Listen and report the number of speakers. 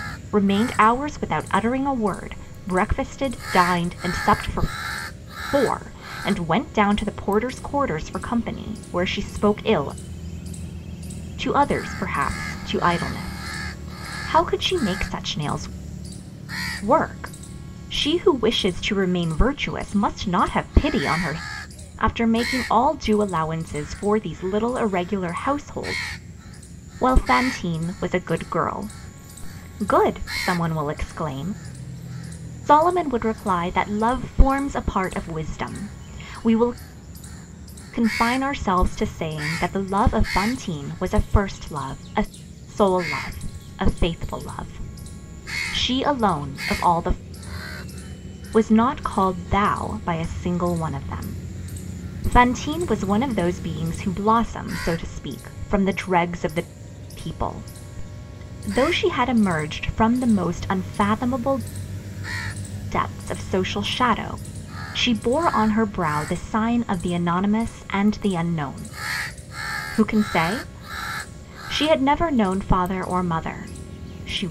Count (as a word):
one